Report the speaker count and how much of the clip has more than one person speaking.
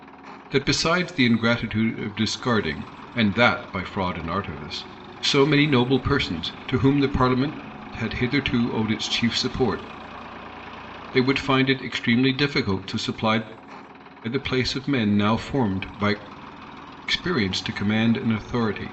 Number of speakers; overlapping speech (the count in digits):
1, no overlap